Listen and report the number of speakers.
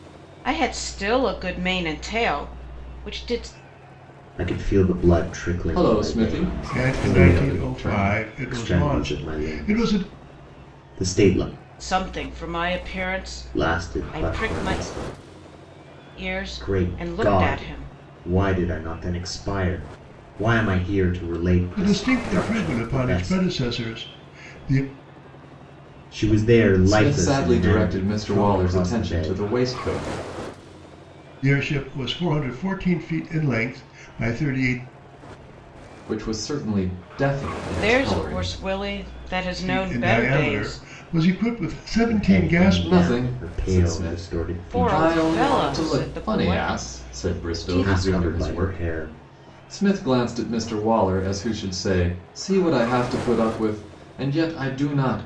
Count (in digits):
4